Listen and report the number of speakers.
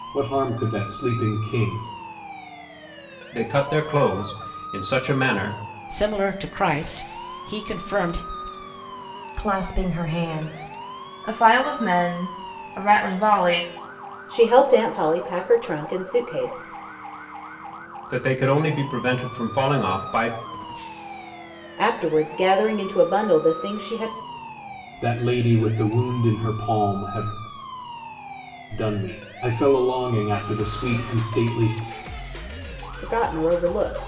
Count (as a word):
six